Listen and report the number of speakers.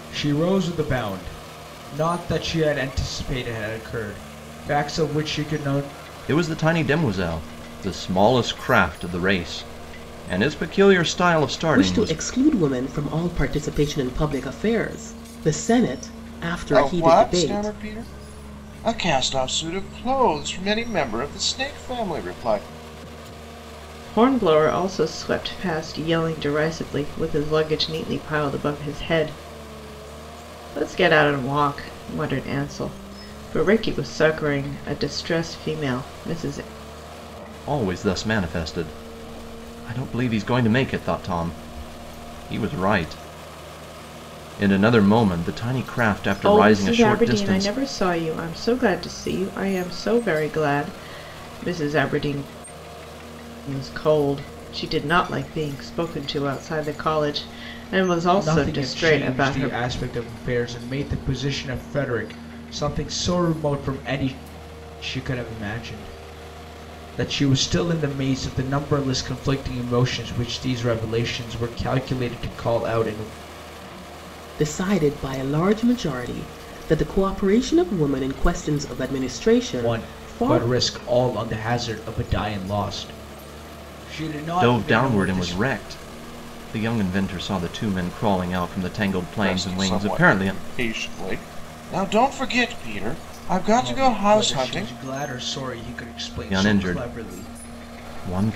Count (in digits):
5